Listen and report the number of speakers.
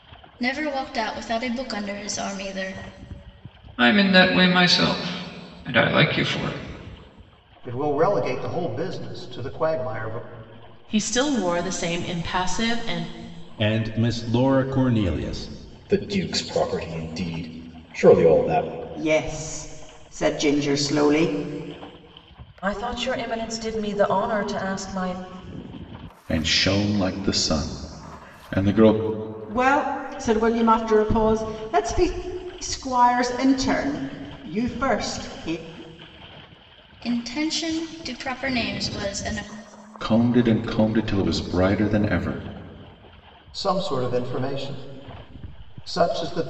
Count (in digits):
9